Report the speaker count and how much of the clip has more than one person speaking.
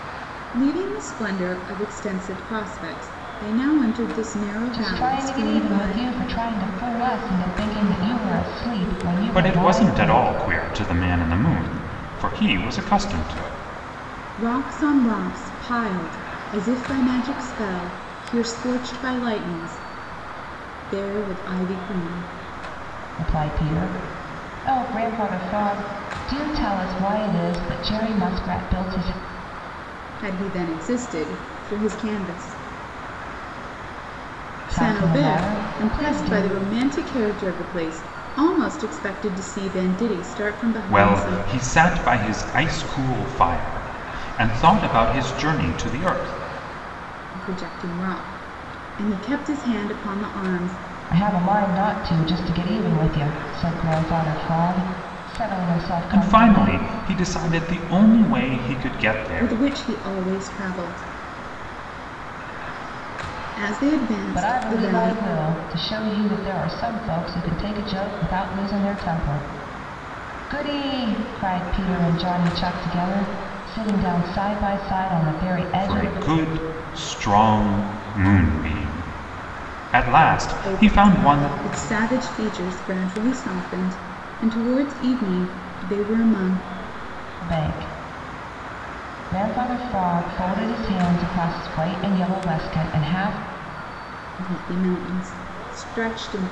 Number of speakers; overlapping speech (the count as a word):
three, about 8%